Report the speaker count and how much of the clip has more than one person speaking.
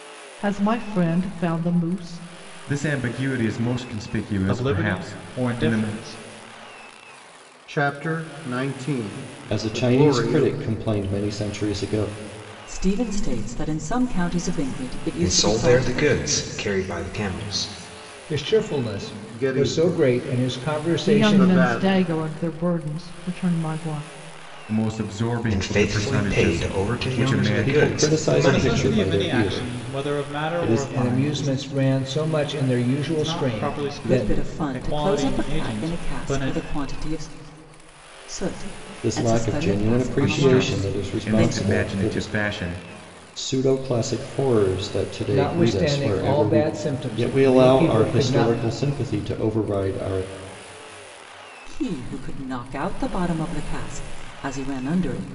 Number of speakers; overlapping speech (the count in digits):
8, about 40%